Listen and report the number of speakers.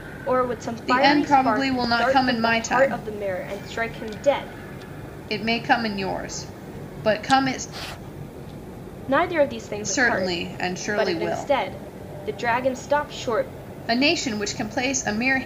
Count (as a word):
two